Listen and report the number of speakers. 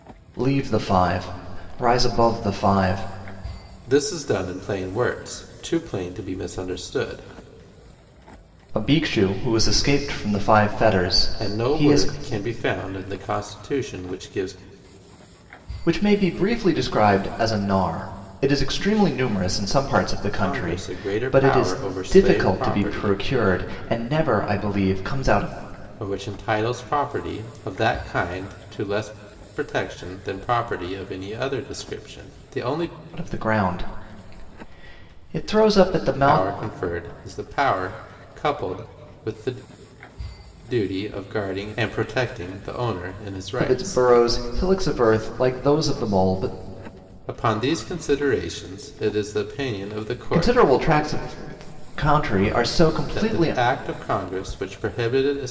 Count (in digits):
2